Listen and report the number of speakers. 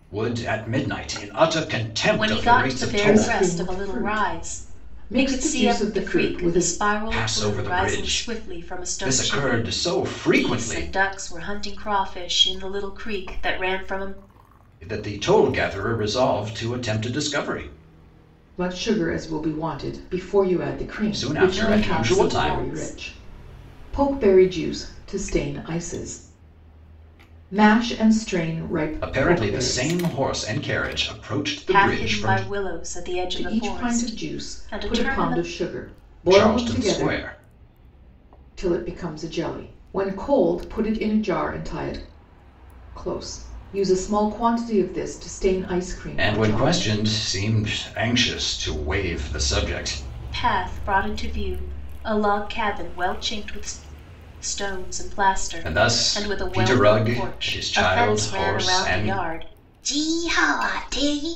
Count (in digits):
3